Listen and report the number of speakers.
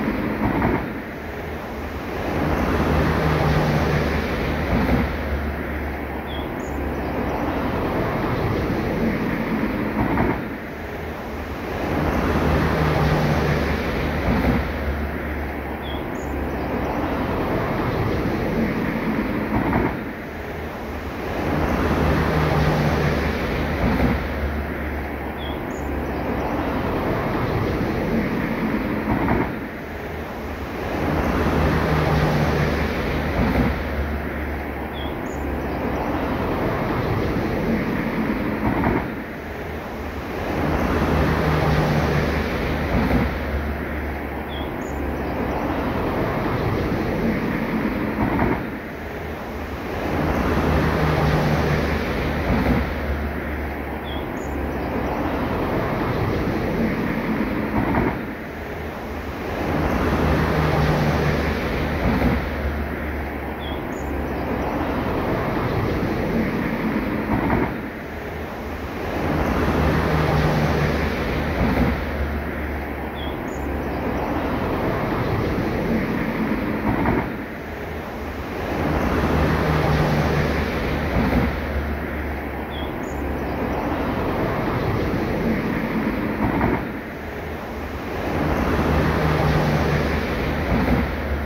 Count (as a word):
zero